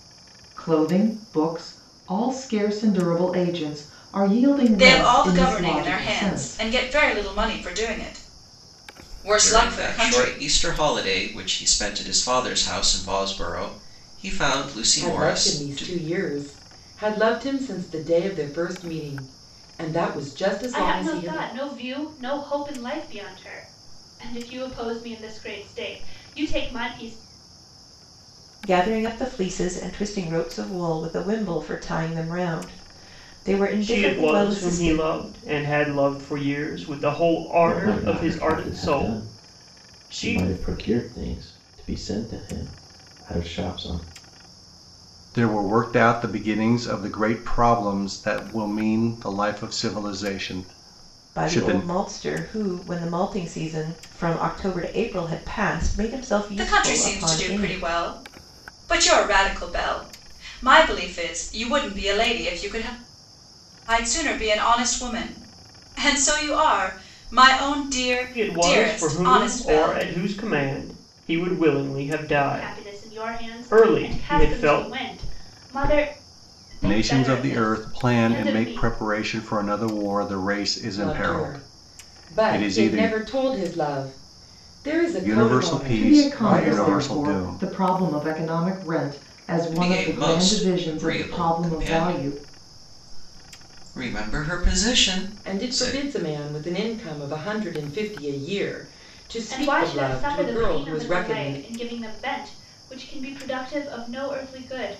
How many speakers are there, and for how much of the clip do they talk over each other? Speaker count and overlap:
9, about 26%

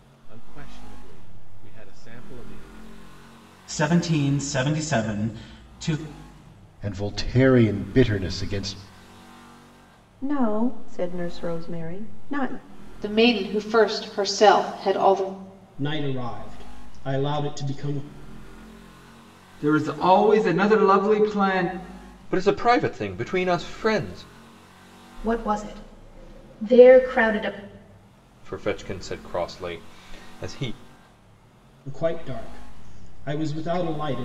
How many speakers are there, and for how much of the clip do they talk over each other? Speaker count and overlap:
9, no overlap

